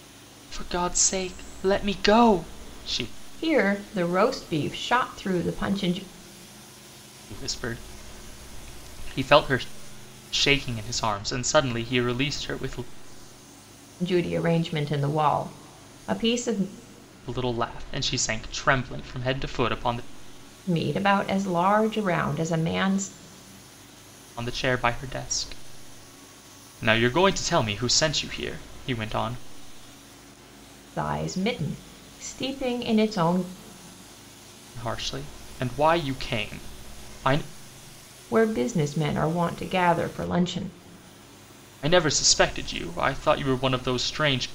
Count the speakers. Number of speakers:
2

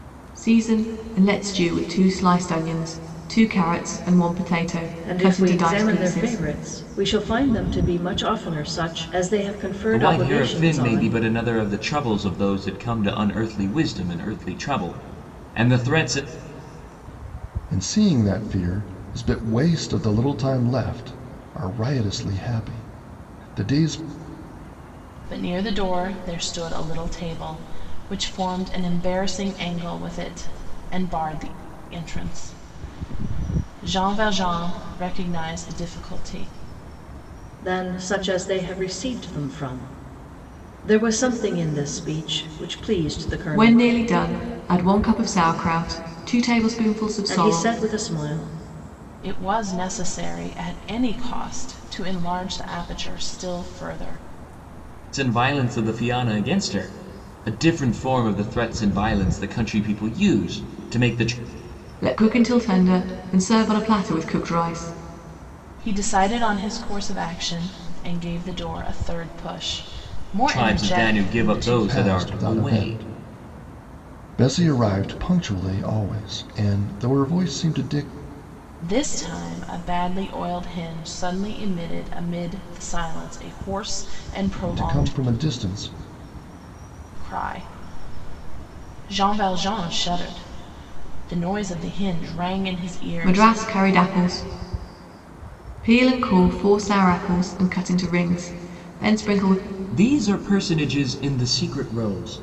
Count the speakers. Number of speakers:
5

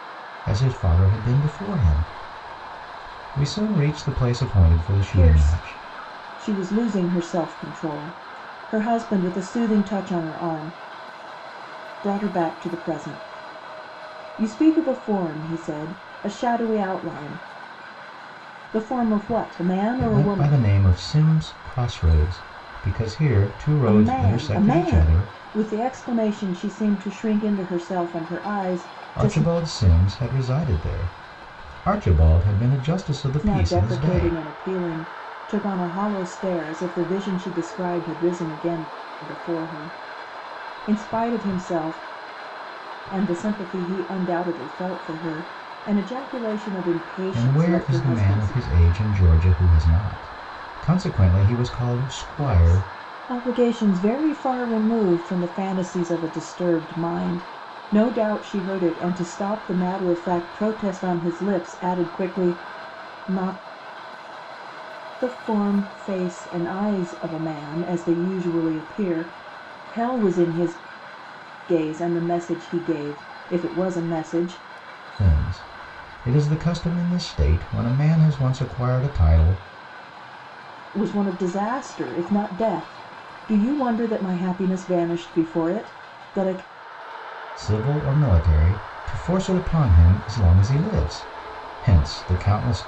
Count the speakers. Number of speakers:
2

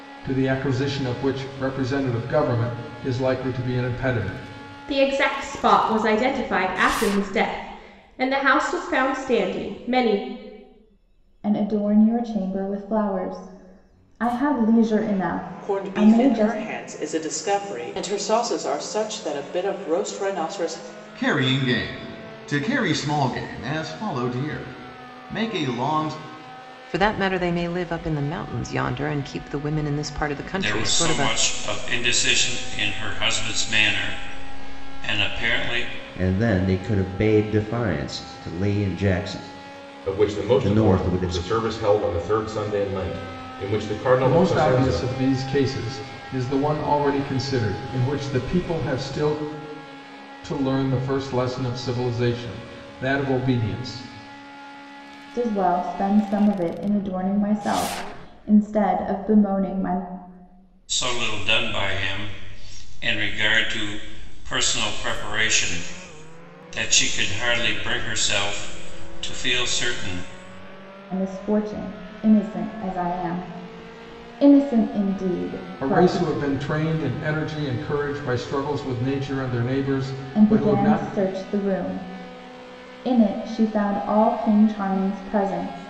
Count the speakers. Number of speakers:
9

